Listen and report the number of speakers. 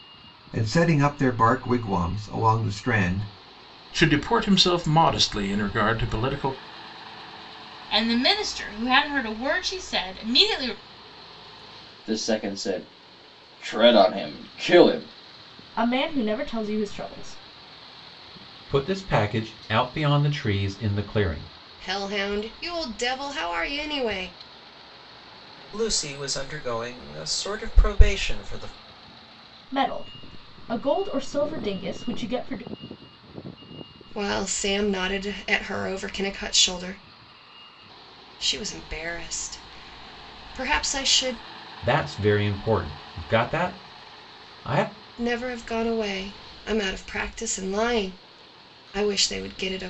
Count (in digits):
8